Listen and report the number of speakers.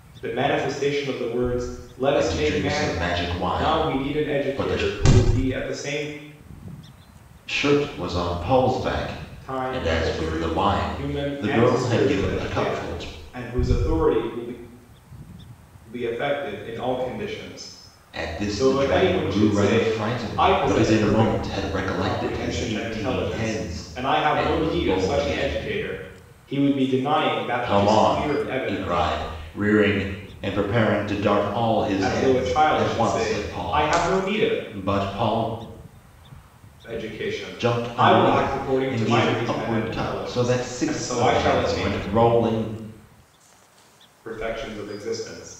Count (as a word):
two